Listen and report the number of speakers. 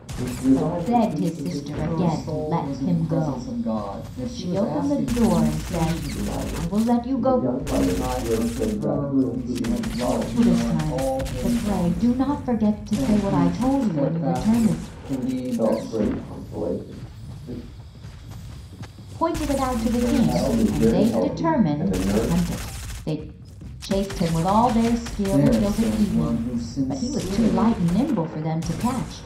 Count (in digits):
3